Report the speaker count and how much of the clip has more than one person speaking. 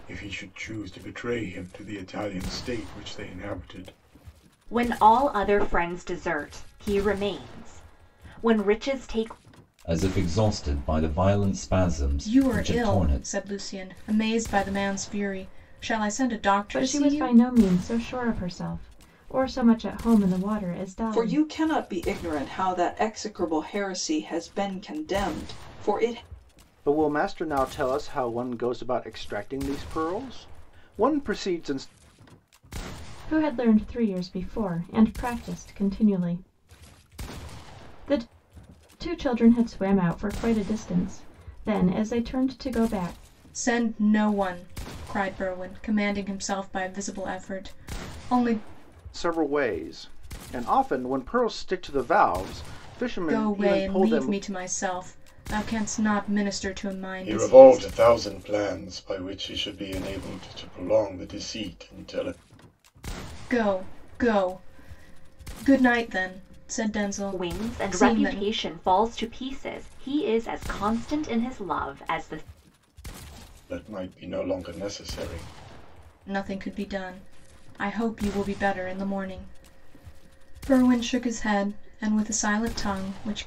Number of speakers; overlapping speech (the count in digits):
7, about 6%